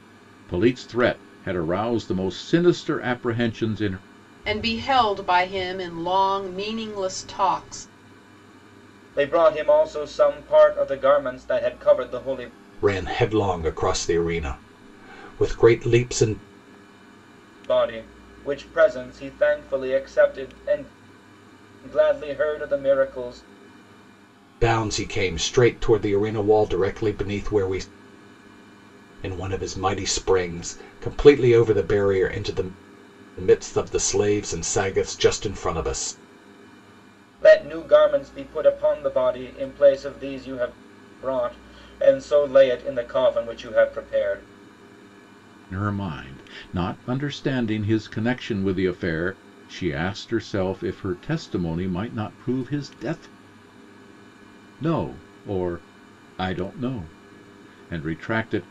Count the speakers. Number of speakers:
4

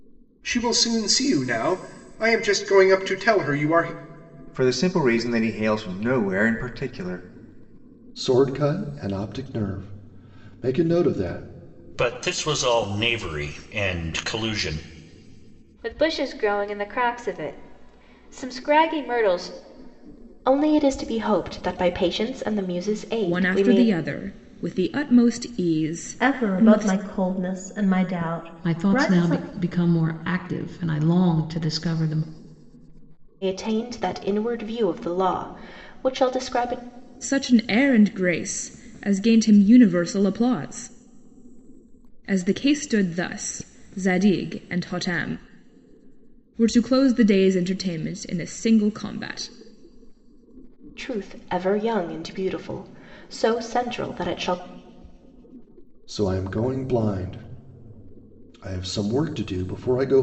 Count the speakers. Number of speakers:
9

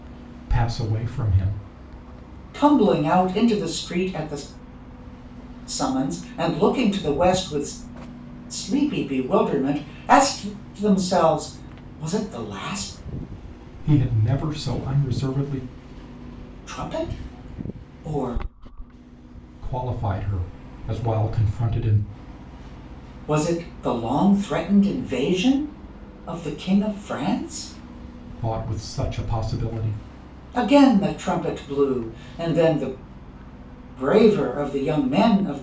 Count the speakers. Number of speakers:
2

